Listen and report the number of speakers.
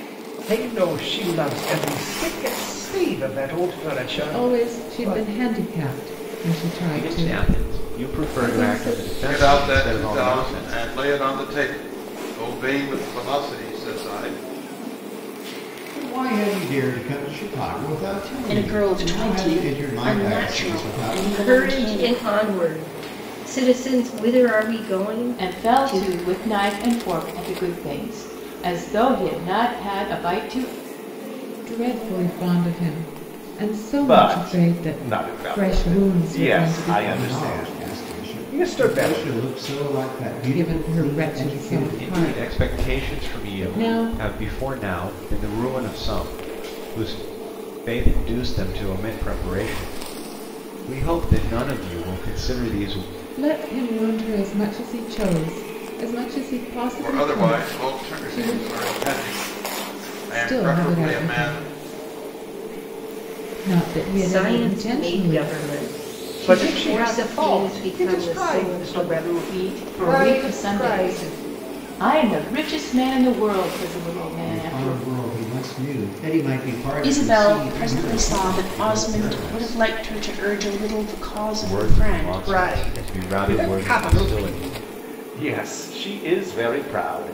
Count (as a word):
eight